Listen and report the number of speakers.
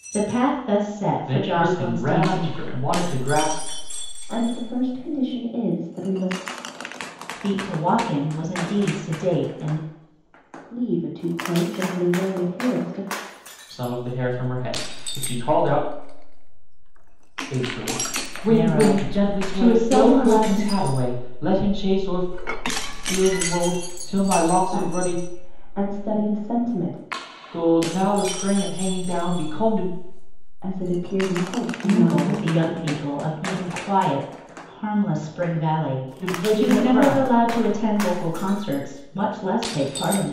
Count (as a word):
three